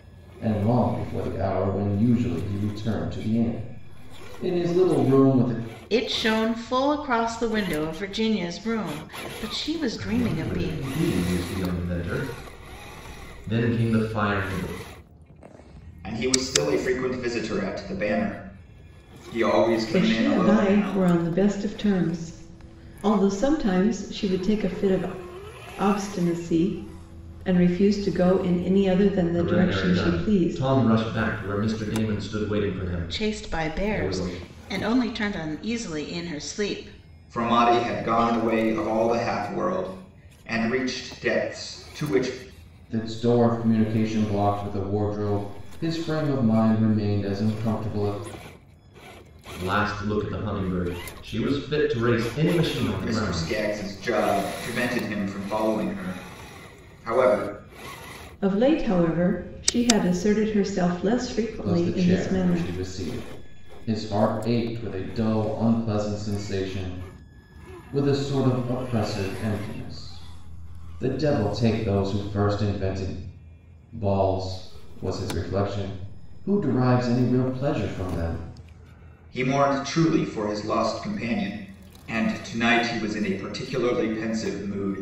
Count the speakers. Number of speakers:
five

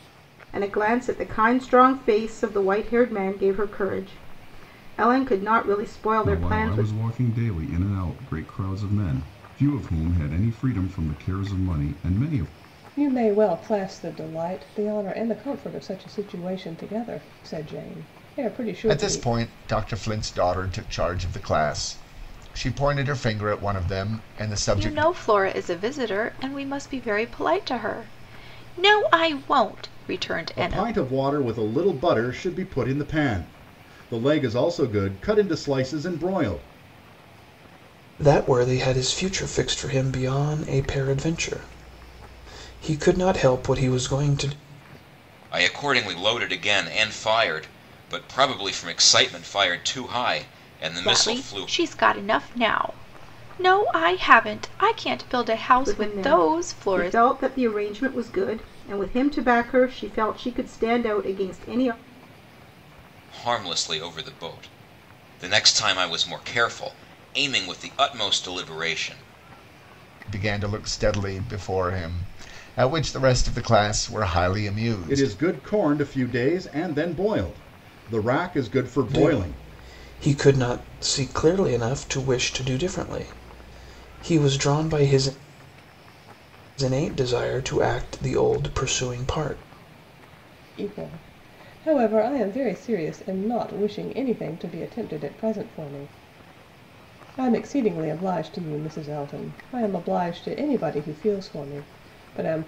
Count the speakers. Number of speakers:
eight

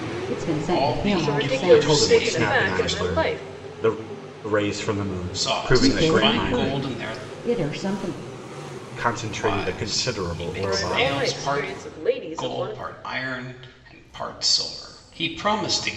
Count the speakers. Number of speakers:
four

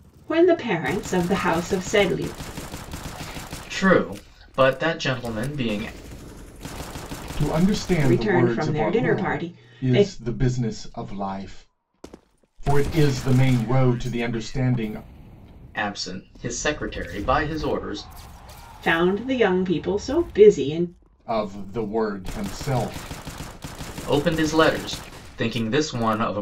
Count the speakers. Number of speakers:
three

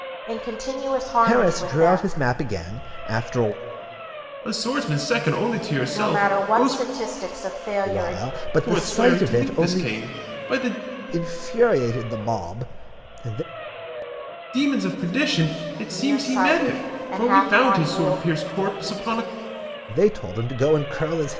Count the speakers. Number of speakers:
three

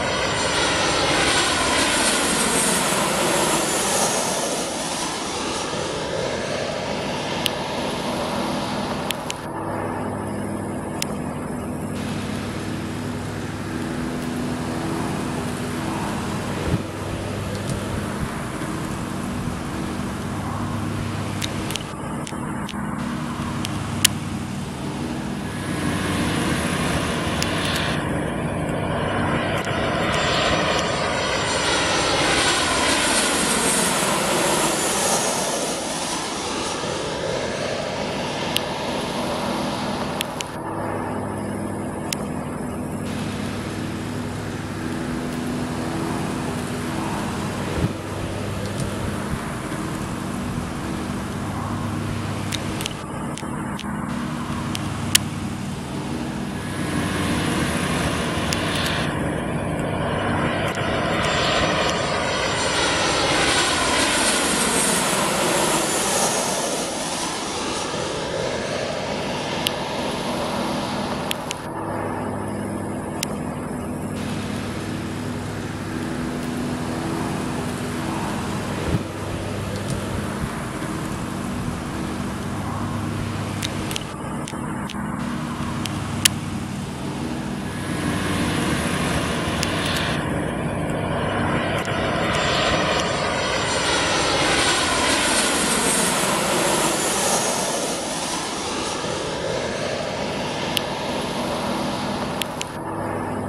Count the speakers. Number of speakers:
zero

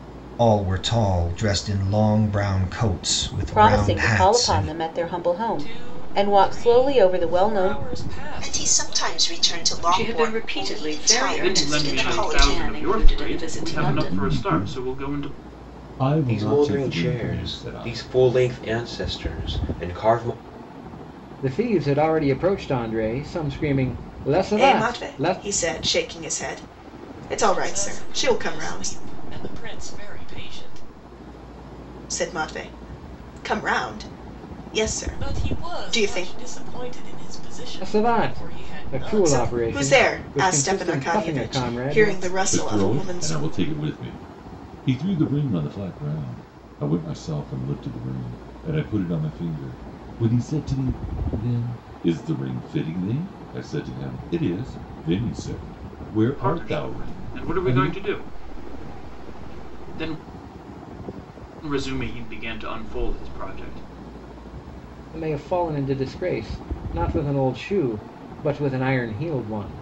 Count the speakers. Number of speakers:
ten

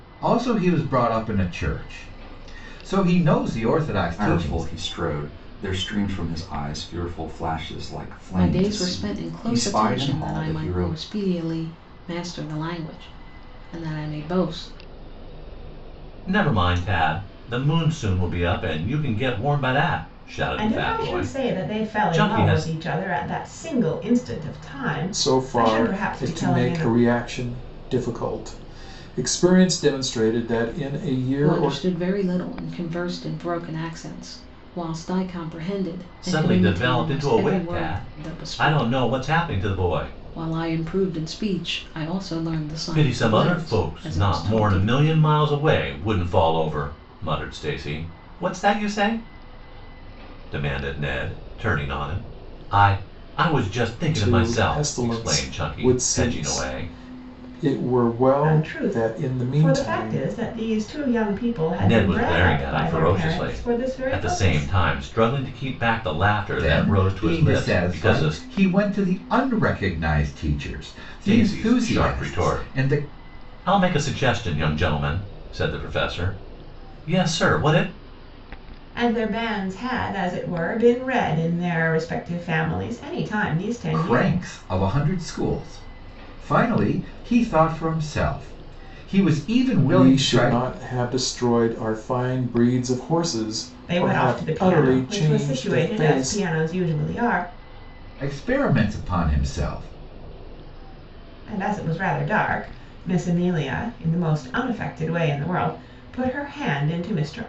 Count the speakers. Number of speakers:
six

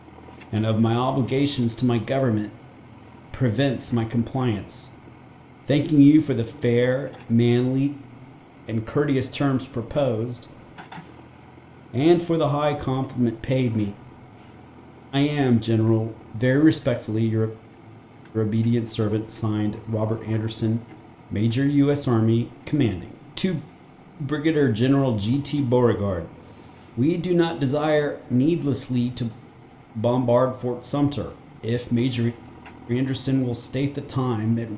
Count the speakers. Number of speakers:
one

